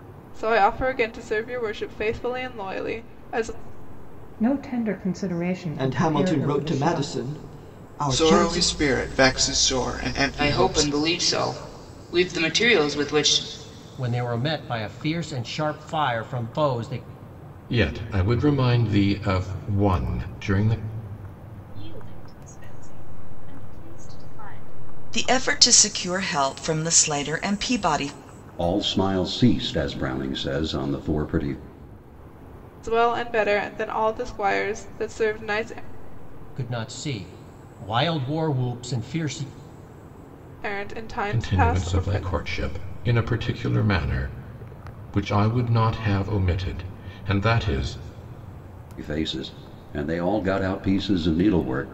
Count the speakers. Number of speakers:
10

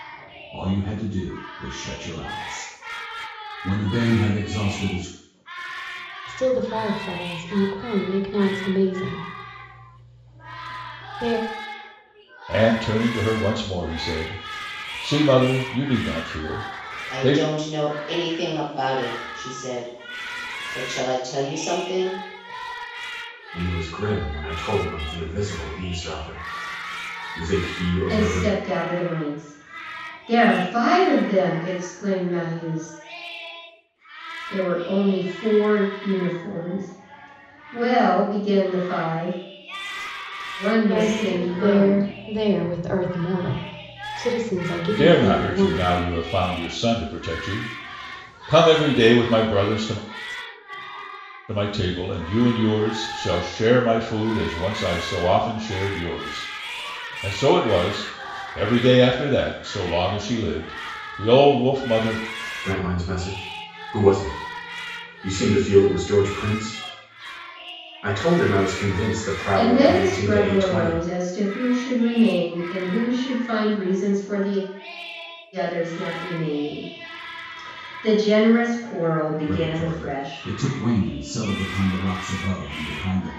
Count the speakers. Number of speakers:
6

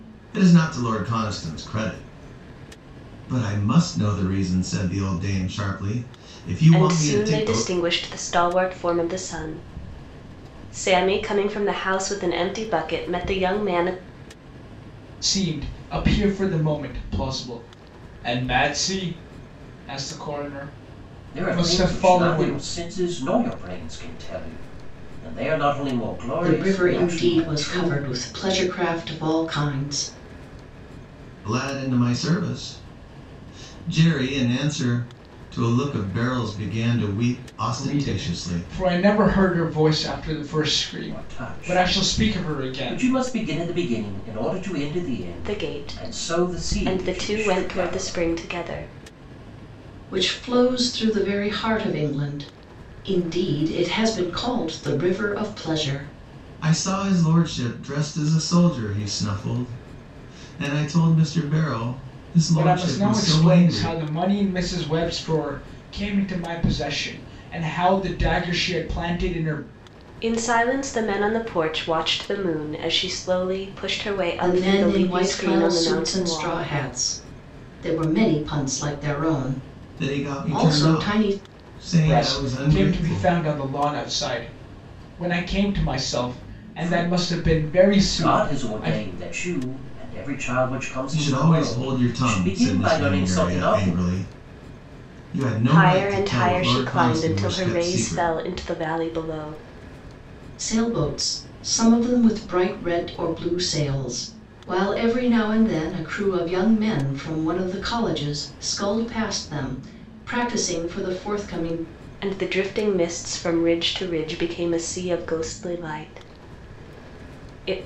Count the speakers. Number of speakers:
5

